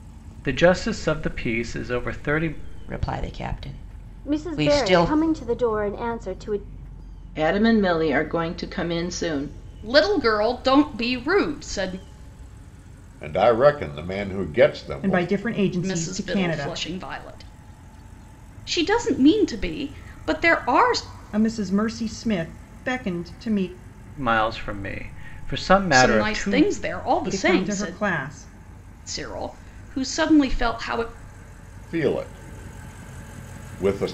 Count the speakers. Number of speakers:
seven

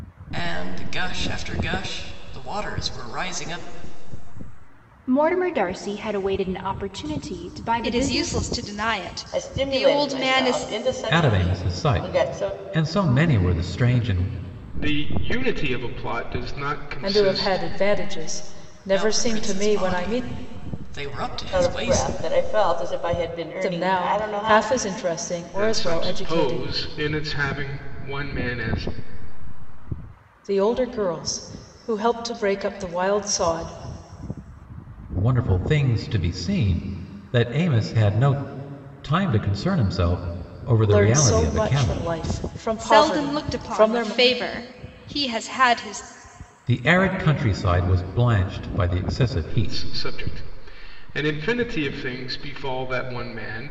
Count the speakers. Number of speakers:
seven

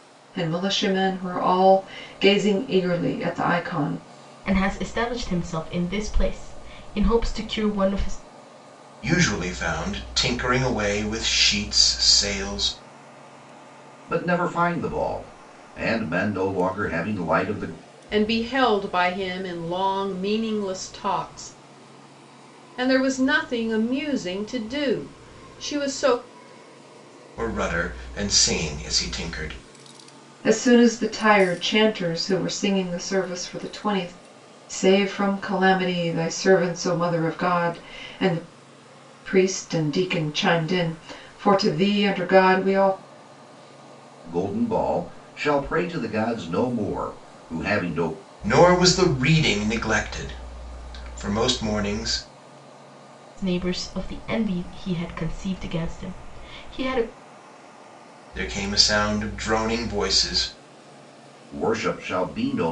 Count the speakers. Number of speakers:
five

